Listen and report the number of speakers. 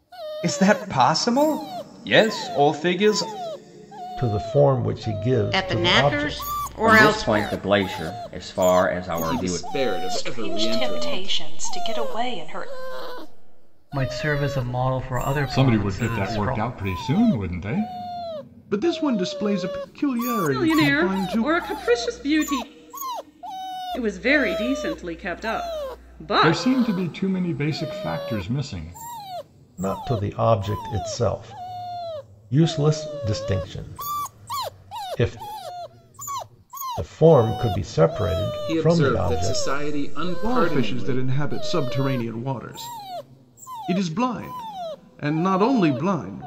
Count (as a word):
ten